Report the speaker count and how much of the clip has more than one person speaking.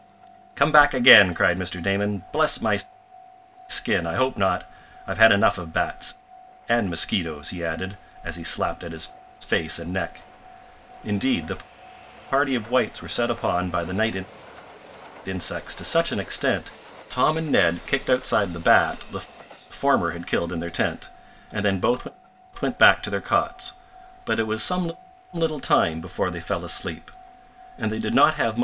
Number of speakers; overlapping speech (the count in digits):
1, no overlap